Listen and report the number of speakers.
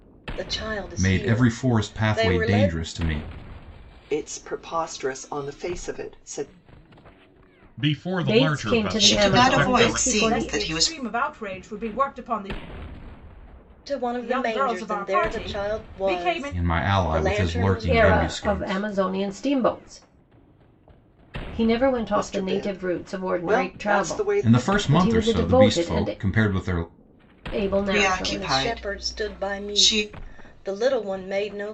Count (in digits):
7